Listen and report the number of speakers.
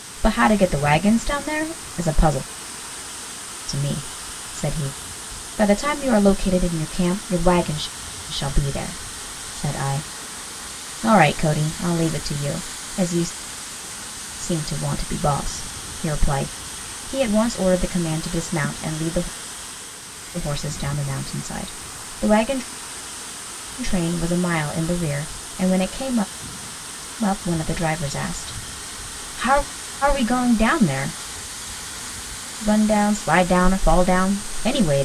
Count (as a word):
one